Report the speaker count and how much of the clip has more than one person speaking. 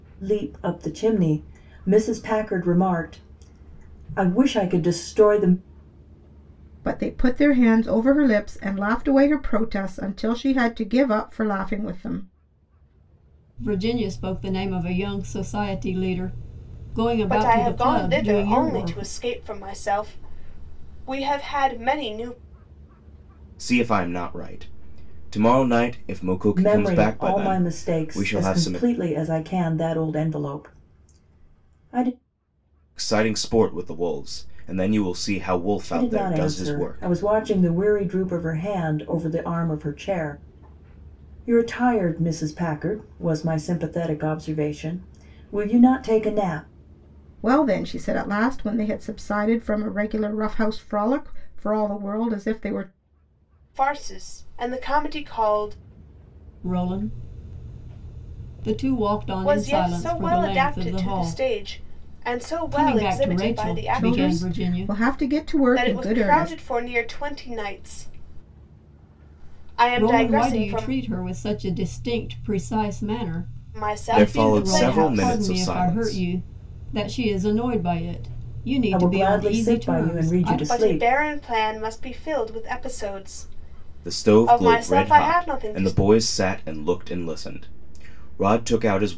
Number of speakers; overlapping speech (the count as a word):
five, about 20%